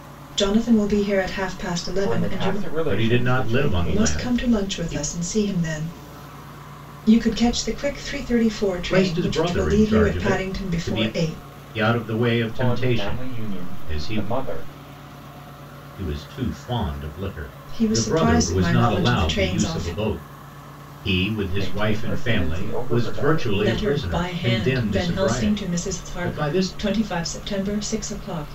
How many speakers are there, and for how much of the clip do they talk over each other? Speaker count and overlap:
3, about 51%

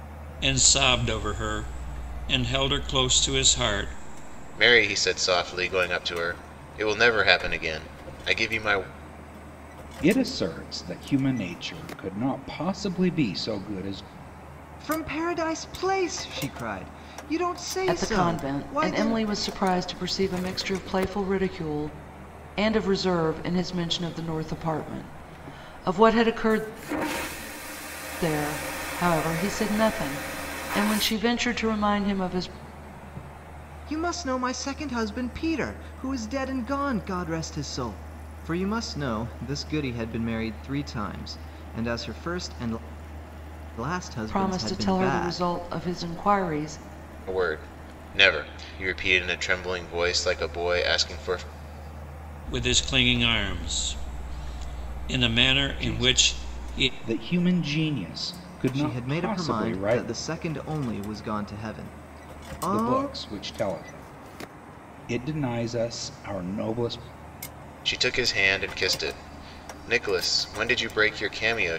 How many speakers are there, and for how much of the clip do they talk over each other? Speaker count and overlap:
5, about 8%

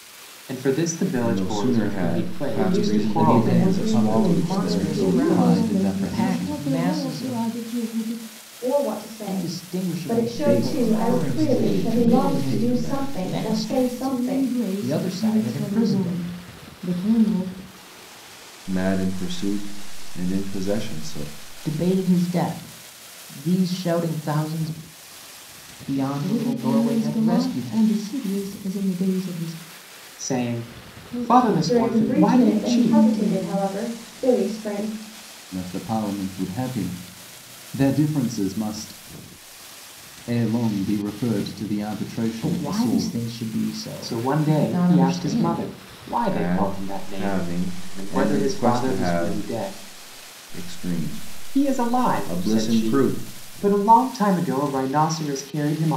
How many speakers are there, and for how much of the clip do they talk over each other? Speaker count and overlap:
7, about 44%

